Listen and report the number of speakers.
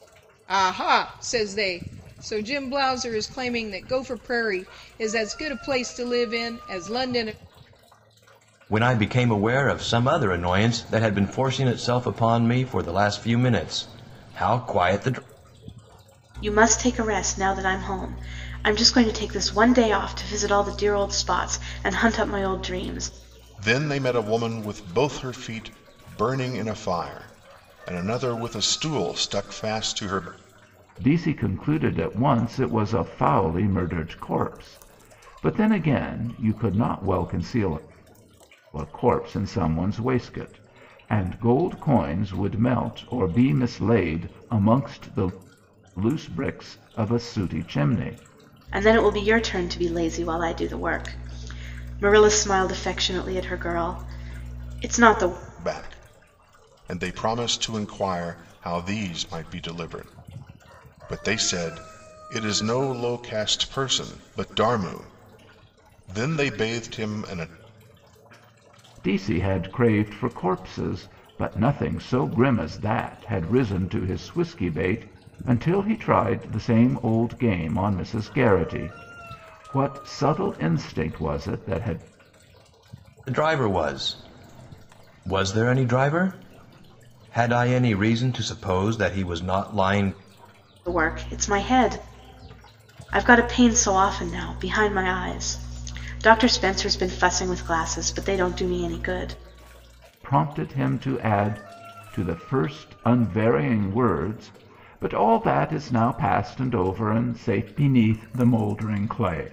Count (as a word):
five